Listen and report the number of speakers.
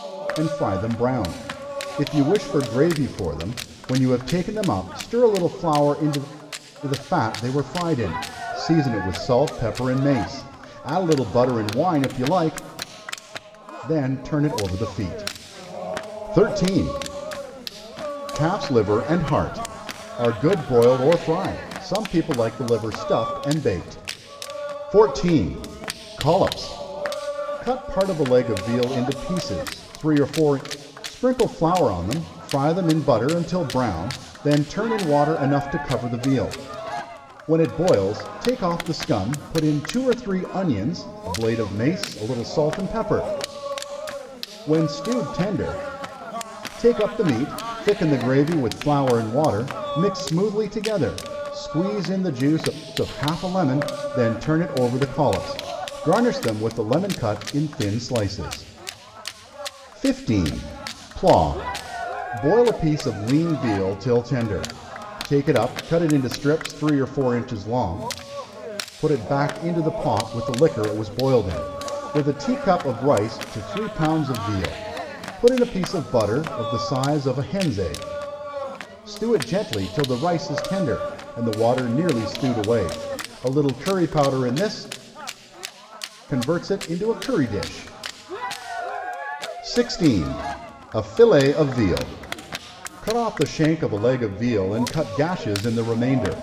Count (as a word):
one